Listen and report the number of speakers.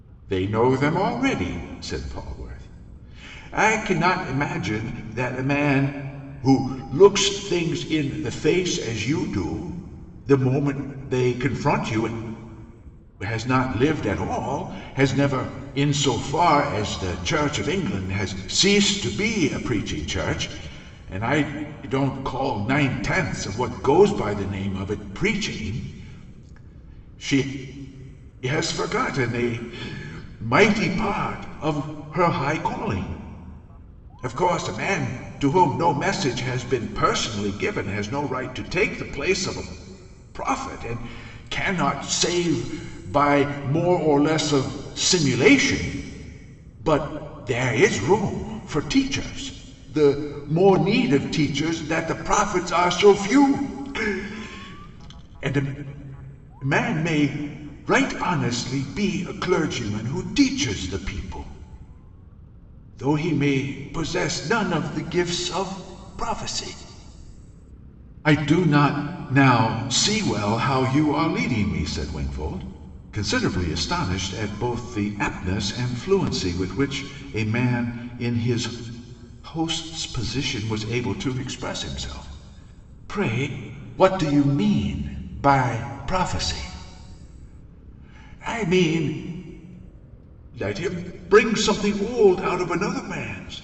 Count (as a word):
one